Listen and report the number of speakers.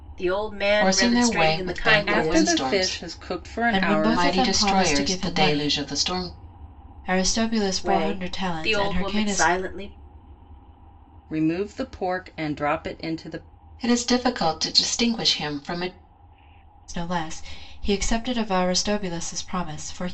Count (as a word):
four